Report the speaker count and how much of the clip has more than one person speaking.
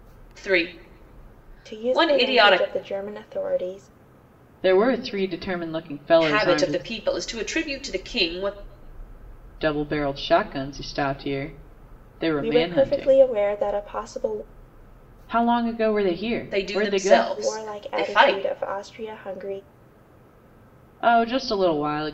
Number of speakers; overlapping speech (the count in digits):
3, about 21%